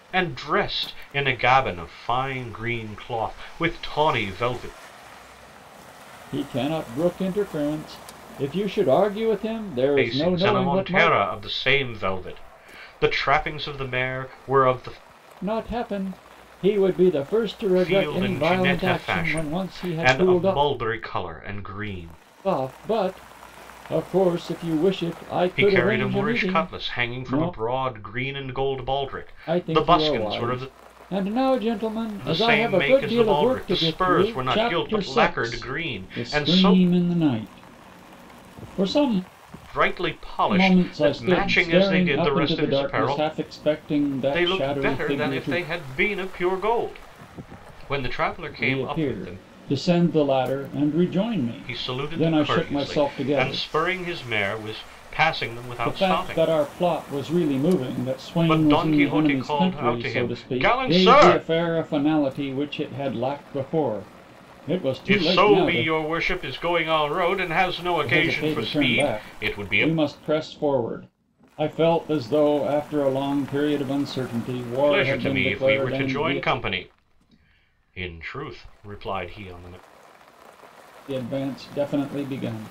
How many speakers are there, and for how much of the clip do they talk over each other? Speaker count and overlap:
2, about 33%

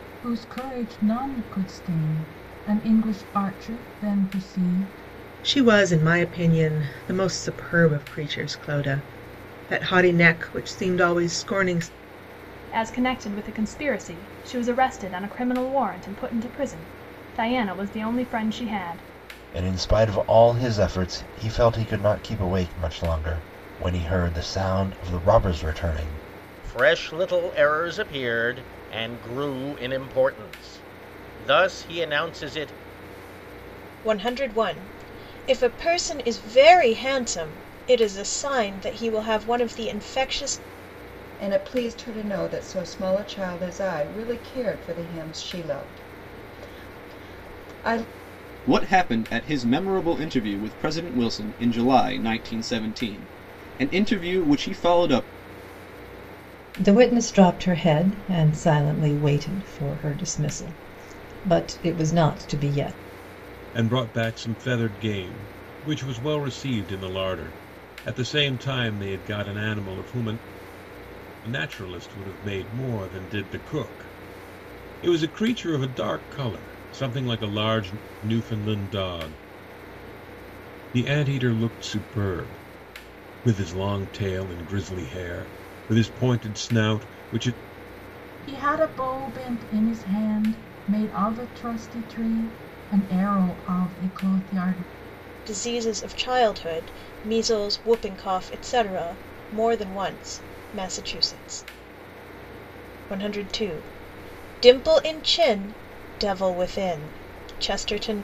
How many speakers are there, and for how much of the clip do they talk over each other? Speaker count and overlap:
10, no overlap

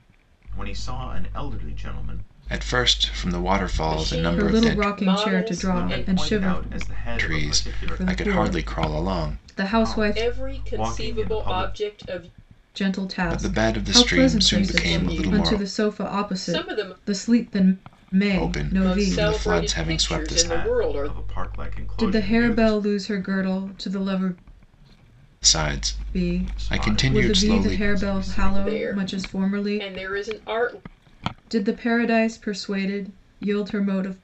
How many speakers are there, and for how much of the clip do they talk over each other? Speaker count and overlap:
4, about 54%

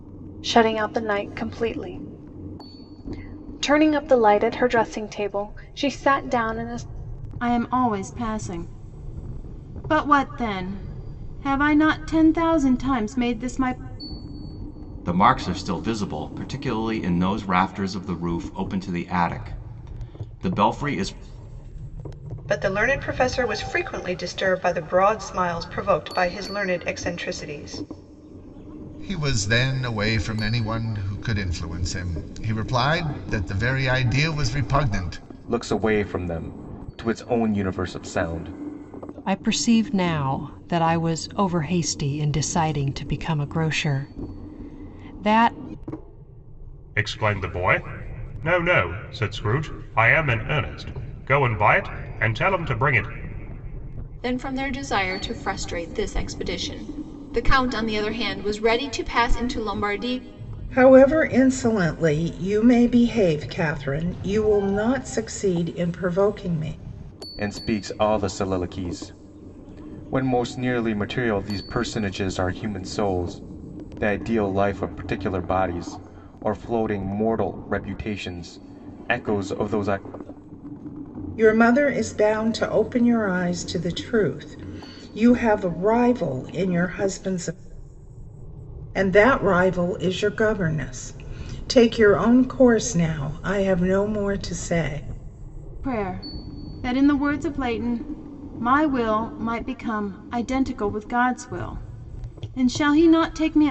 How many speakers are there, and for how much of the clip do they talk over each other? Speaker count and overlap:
10, no overlap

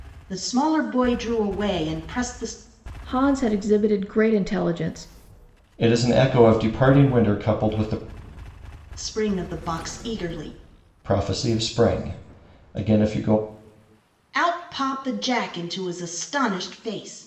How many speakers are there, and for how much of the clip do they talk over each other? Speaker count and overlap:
3, no overlap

